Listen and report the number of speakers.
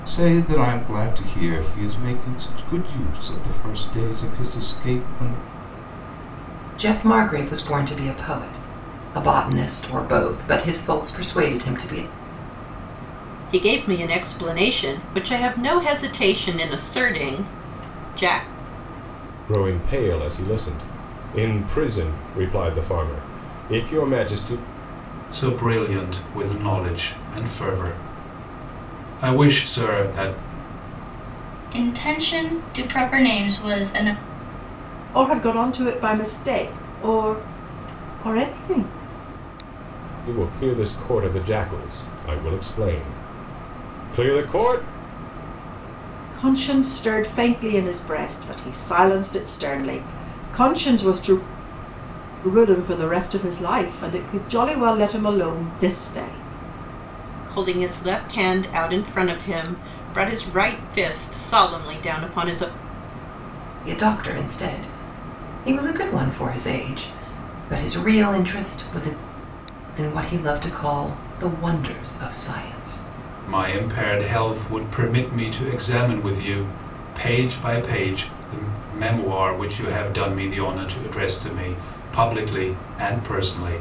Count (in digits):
7